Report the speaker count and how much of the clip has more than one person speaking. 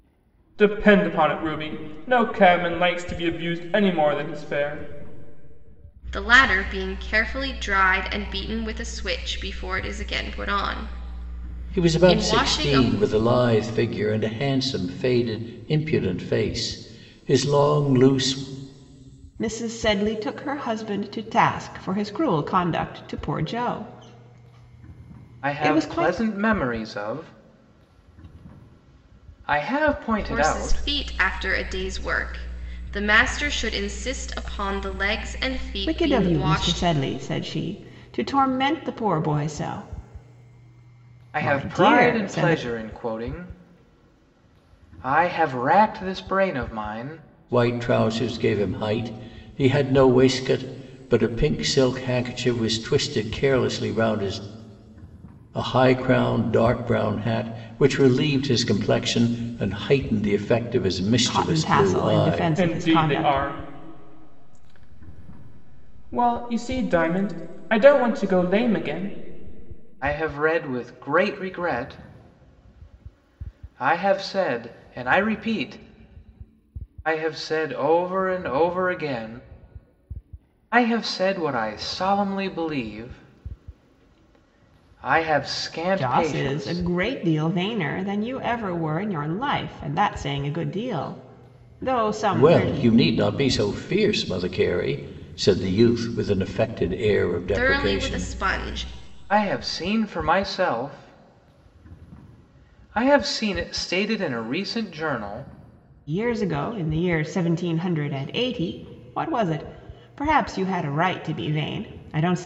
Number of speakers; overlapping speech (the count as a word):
five, about 9%